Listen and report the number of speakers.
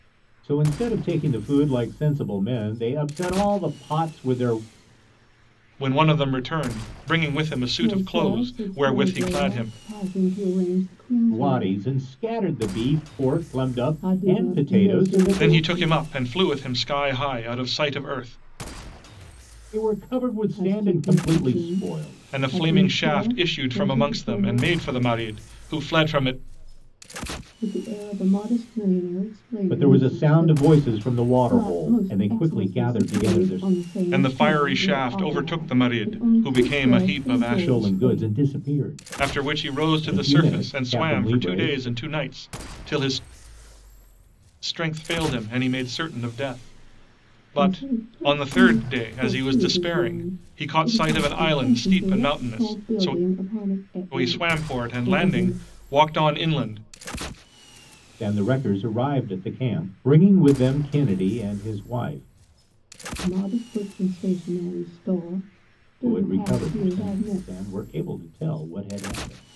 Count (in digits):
3